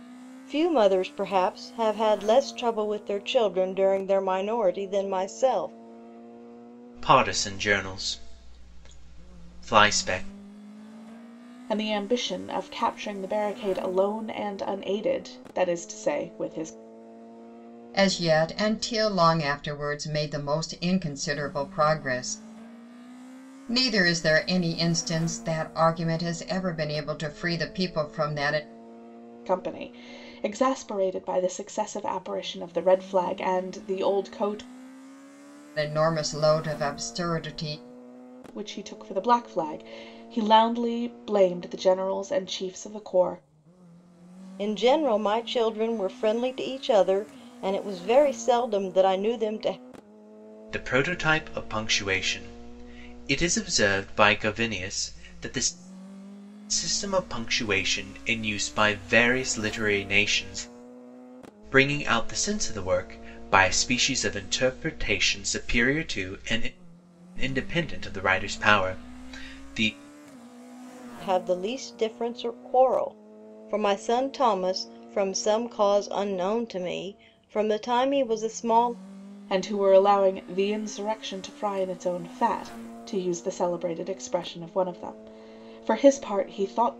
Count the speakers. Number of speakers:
4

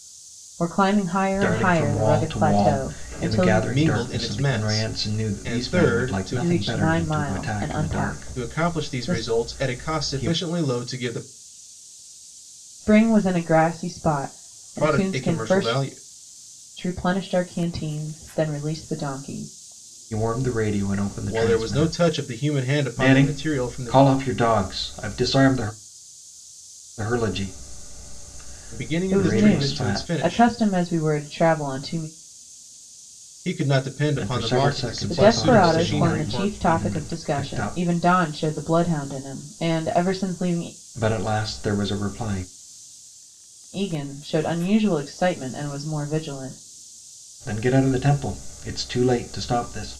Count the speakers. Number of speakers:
3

